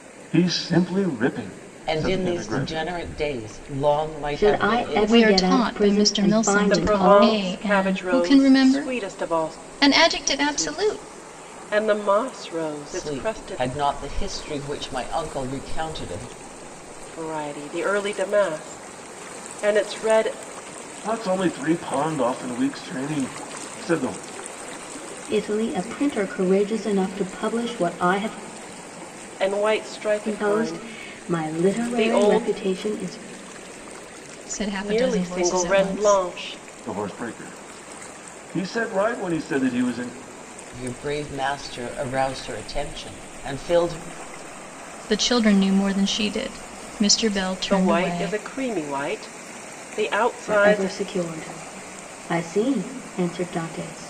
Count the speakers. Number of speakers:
5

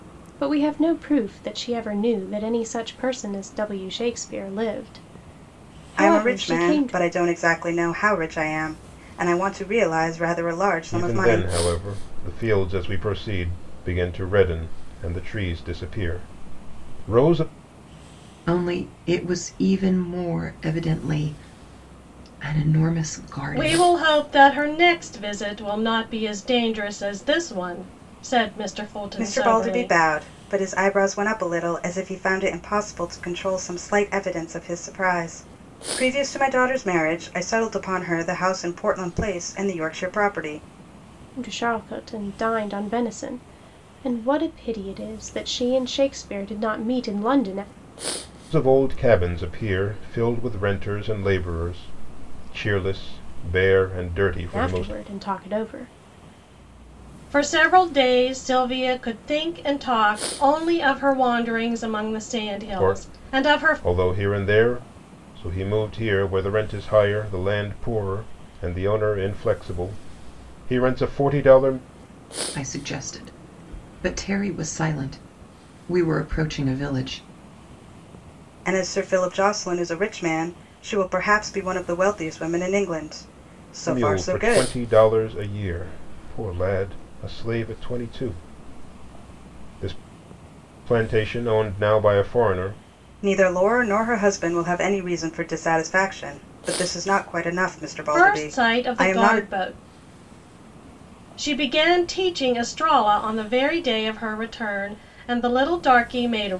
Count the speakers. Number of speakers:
5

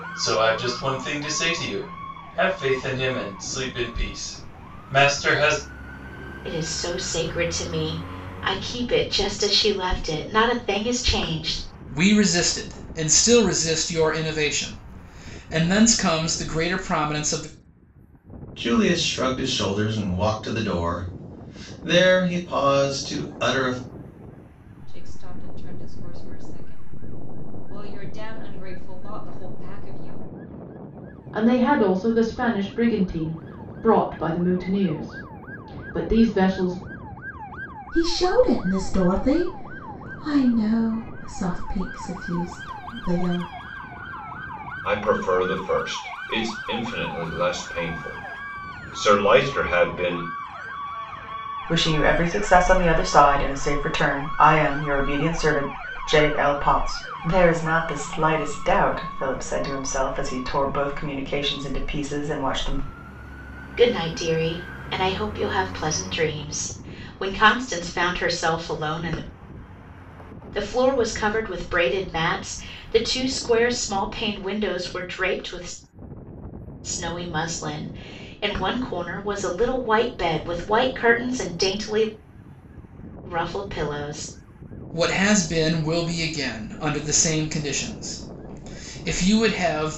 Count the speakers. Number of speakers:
9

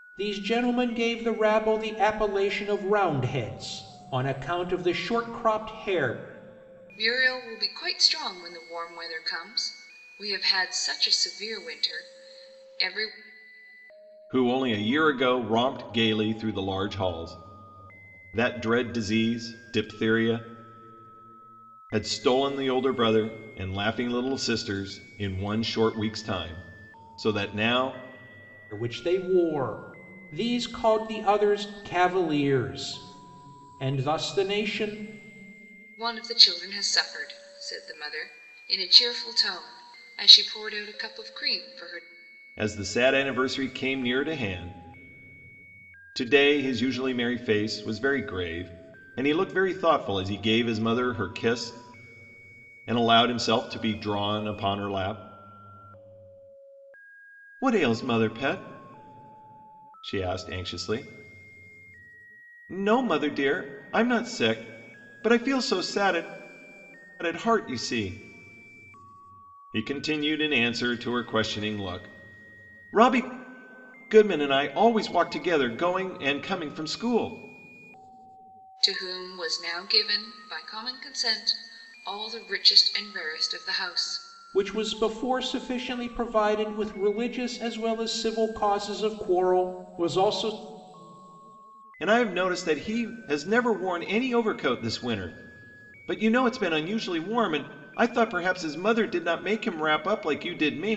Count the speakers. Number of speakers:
3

